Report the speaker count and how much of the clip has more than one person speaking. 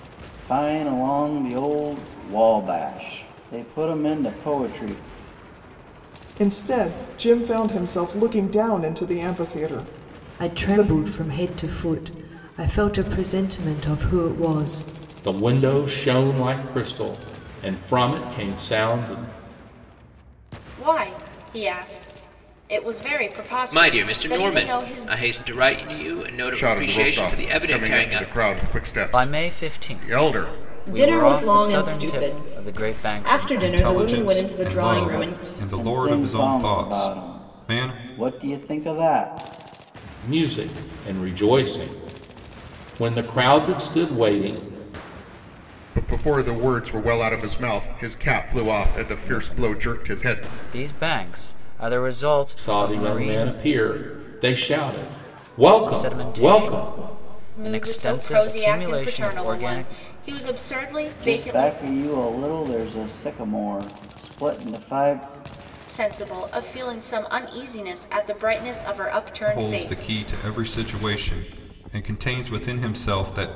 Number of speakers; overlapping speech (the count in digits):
10, about 26%